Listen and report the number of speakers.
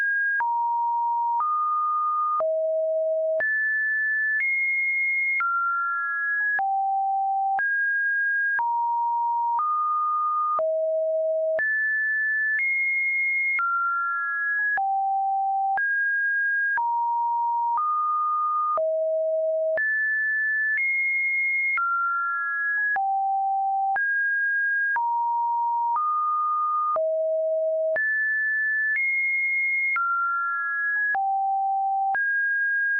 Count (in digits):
0